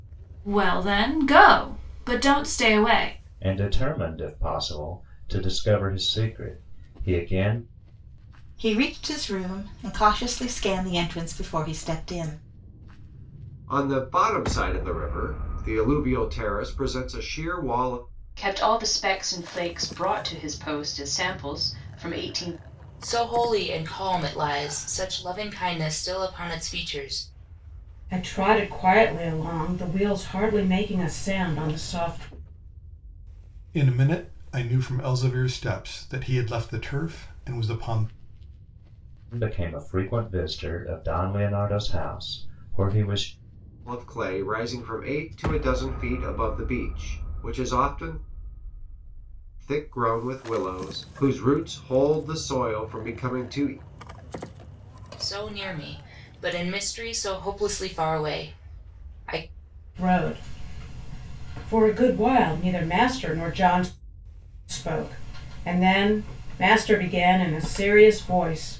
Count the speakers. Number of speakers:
8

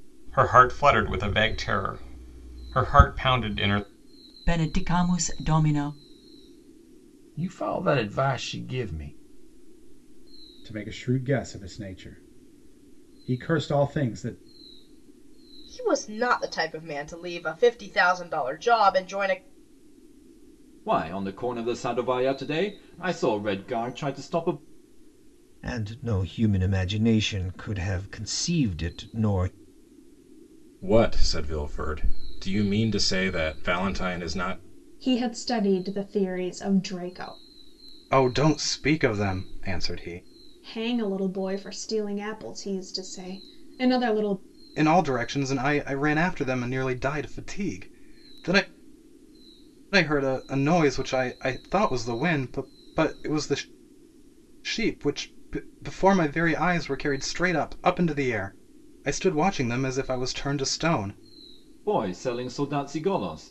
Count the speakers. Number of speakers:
10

